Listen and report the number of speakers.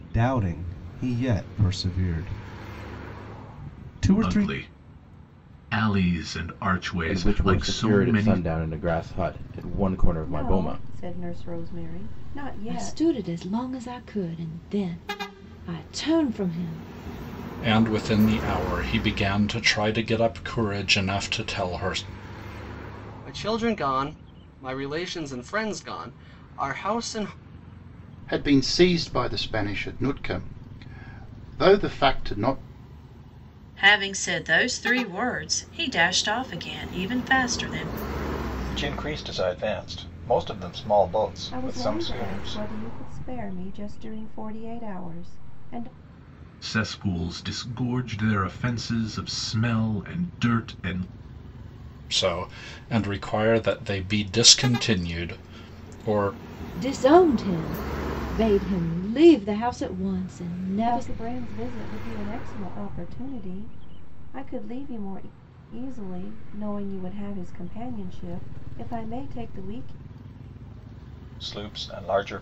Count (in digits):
10